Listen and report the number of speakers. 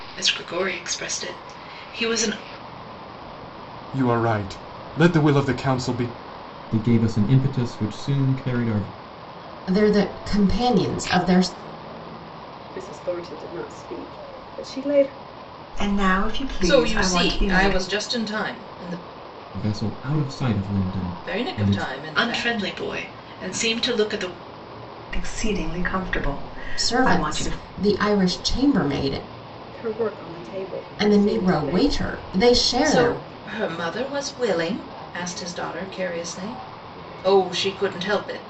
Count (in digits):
7